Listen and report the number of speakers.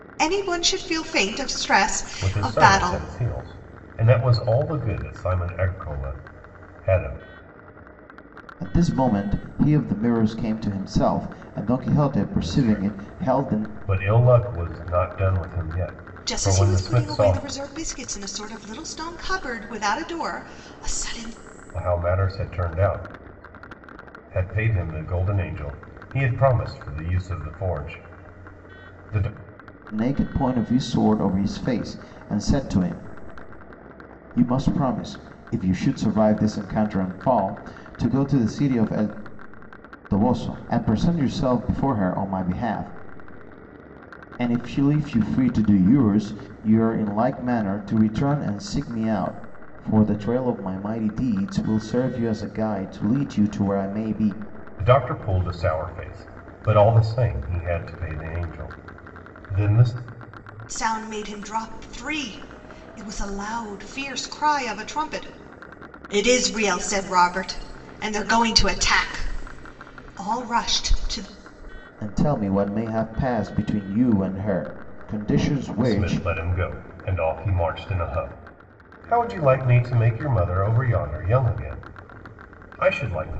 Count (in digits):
3